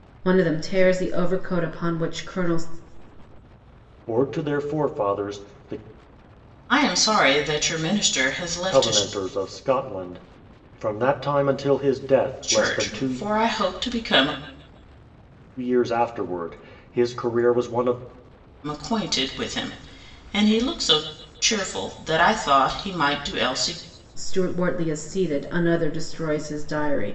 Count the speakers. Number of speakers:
3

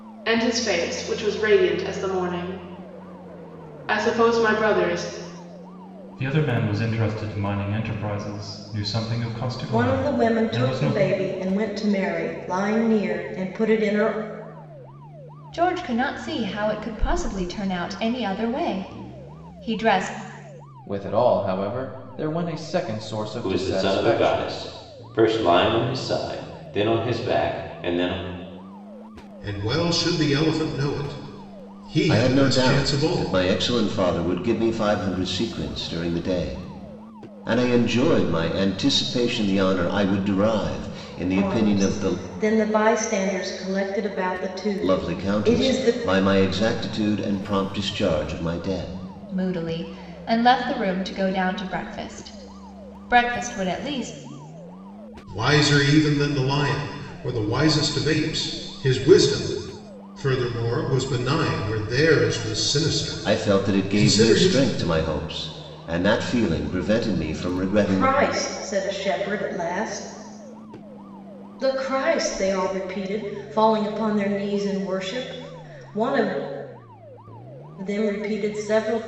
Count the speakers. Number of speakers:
8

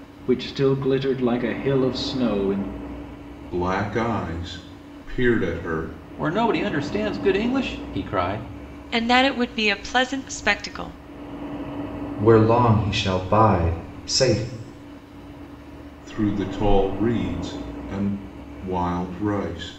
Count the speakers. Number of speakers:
5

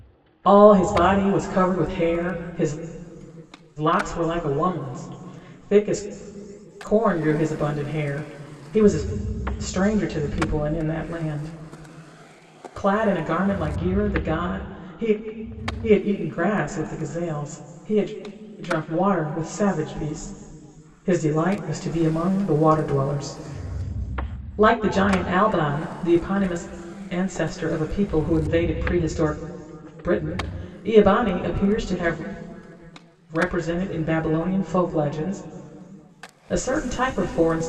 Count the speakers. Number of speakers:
1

